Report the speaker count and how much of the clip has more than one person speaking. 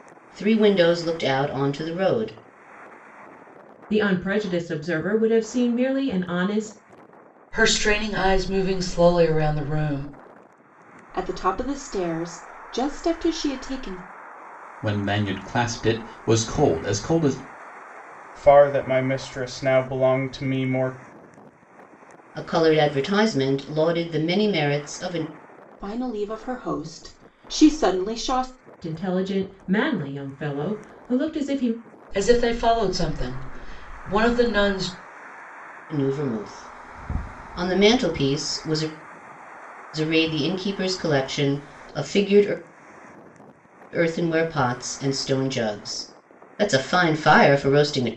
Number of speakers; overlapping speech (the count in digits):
6, no overlap